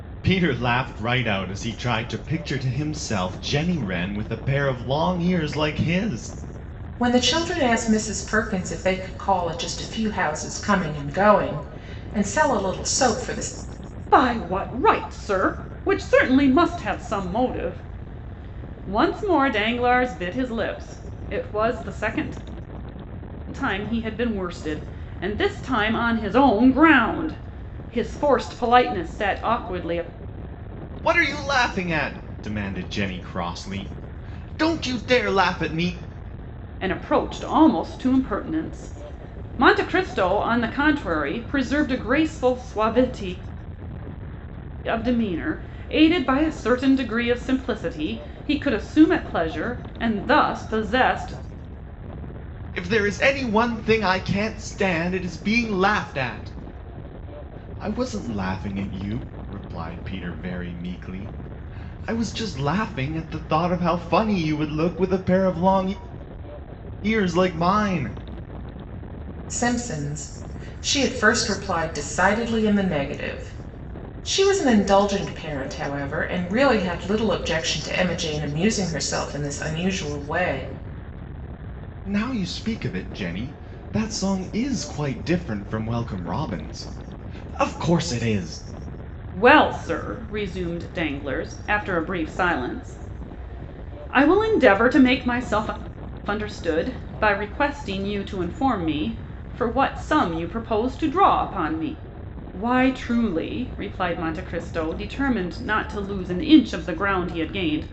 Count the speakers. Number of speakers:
three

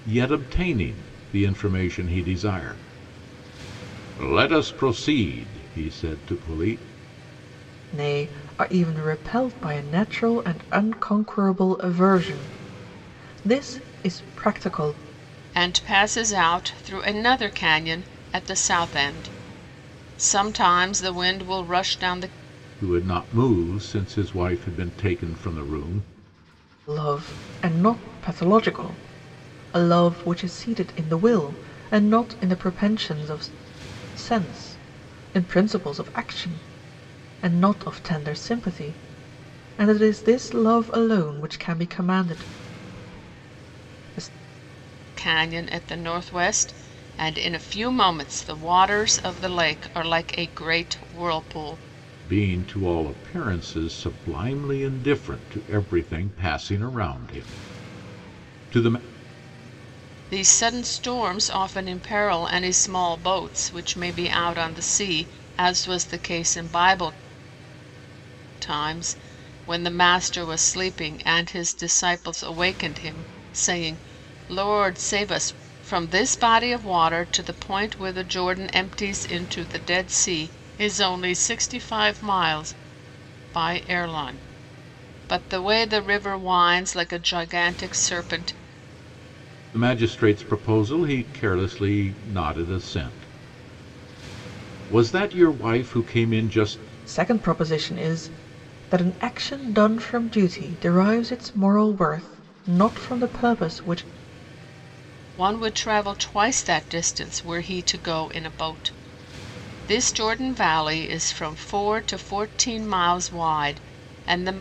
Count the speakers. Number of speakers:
three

